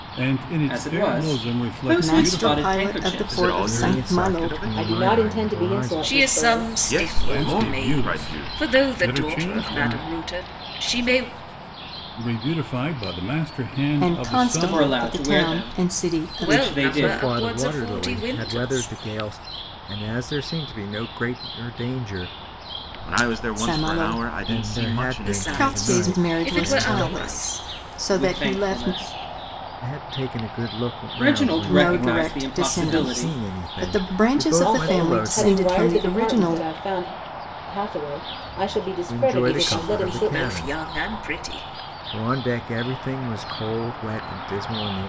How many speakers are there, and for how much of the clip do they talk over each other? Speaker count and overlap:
seven, about 58%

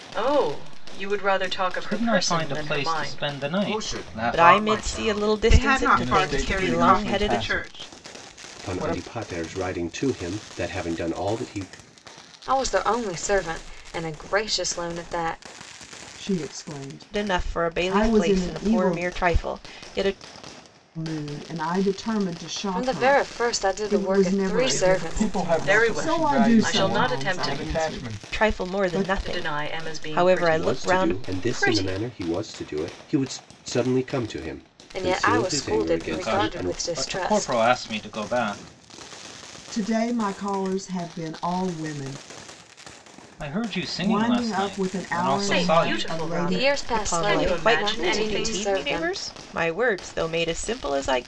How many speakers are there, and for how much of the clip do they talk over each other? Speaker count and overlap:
nine, about 49%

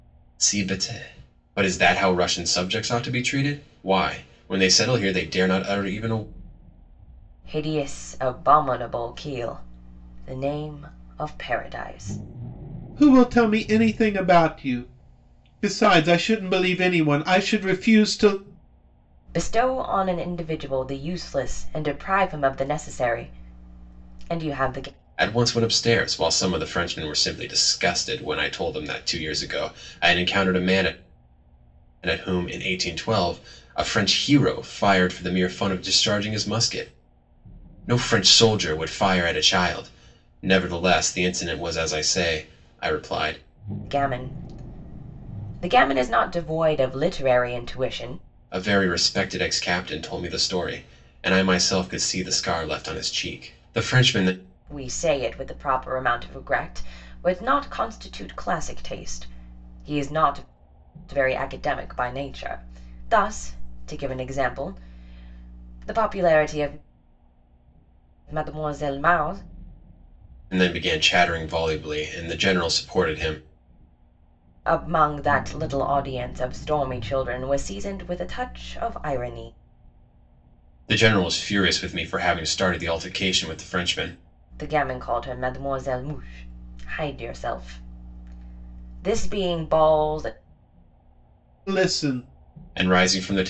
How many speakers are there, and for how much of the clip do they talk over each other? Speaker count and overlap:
three, no overlap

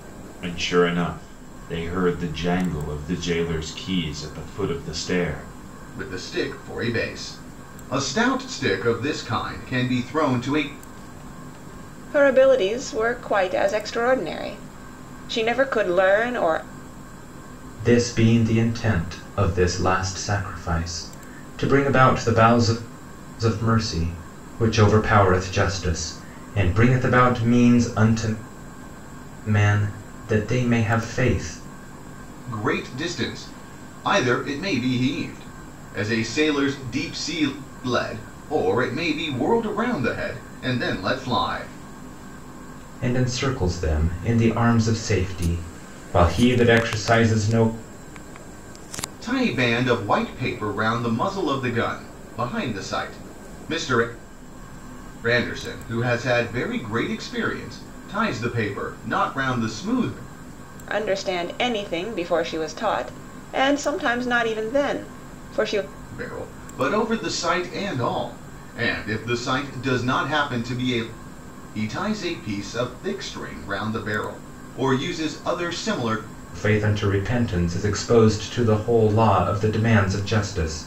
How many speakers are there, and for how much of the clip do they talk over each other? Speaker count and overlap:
four, no overlap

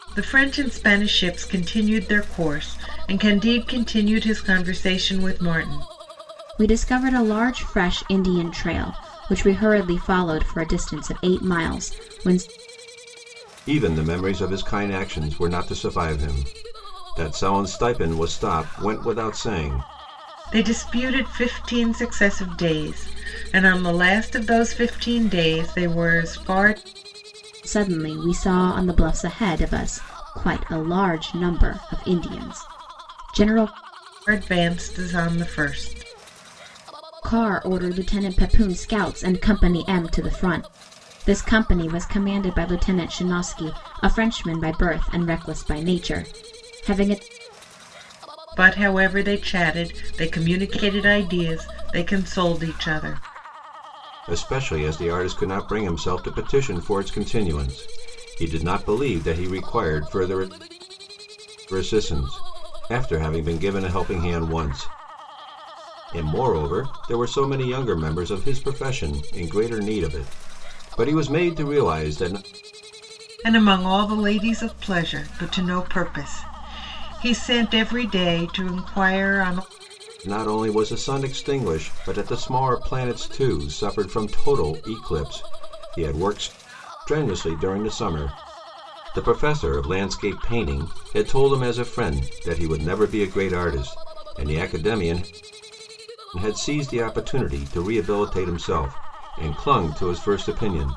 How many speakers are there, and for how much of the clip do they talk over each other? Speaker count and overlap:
three, no overlap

